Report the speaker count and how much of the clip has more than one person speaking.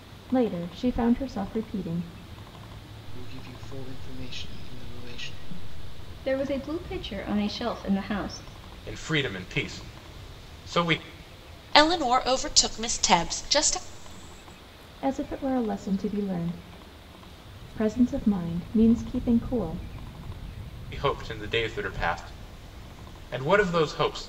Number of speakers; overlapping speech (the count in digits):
5, no overlap